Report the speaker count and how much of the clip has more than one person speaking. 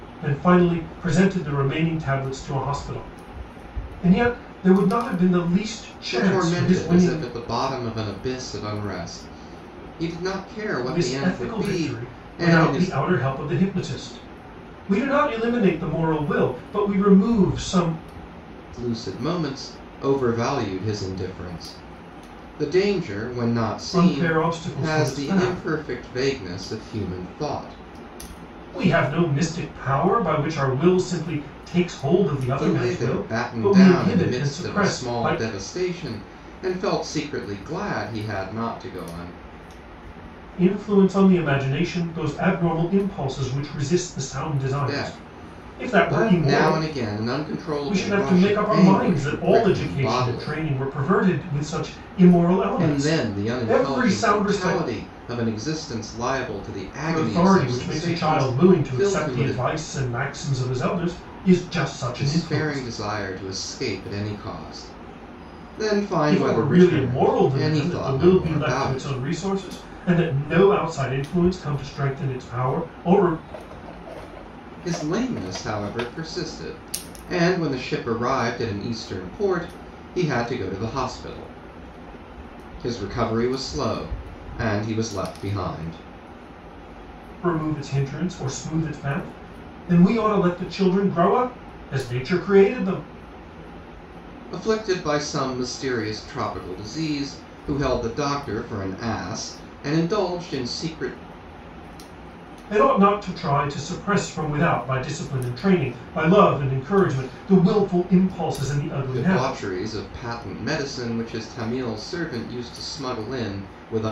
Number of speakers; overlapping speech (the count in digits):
2, about 19%